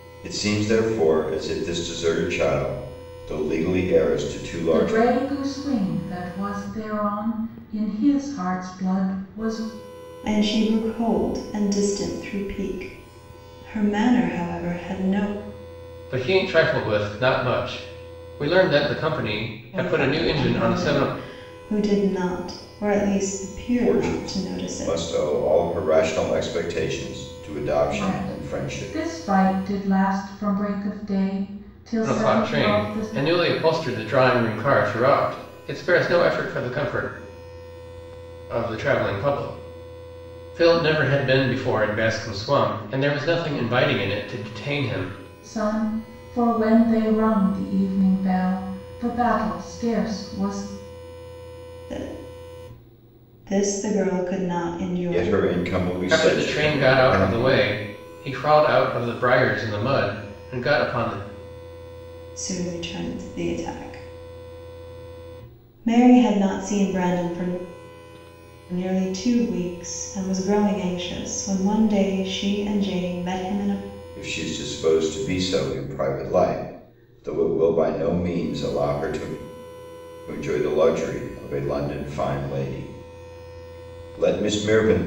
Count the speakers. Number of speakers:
four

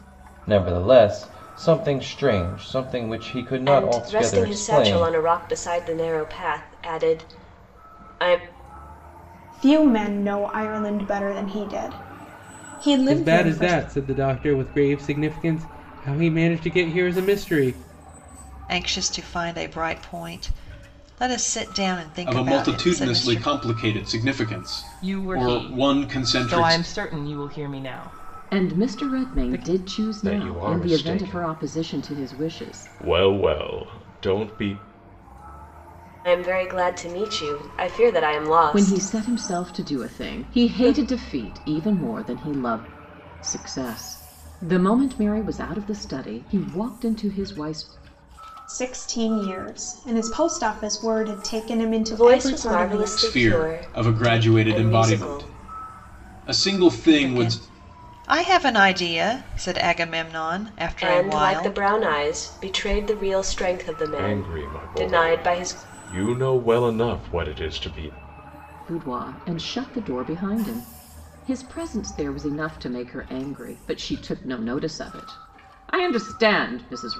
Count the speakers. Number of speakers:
nine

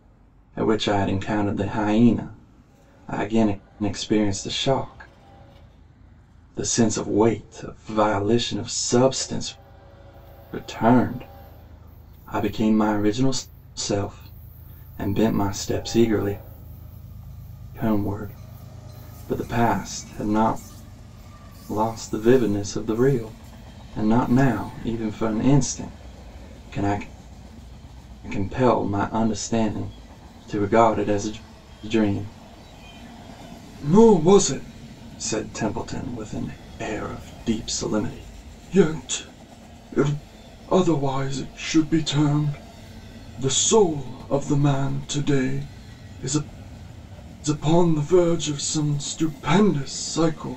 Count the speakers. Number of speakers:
one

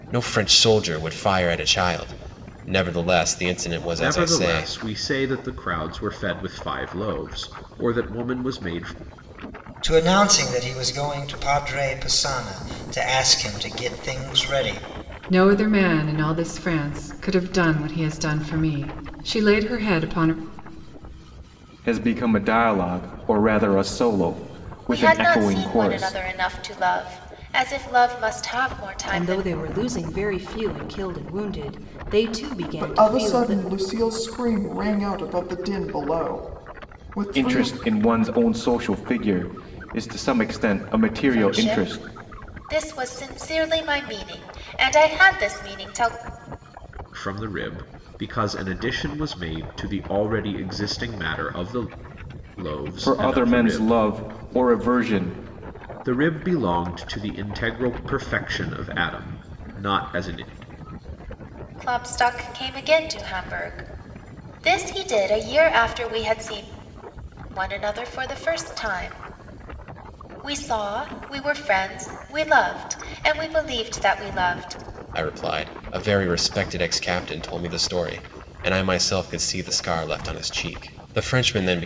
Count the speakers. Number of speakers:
eight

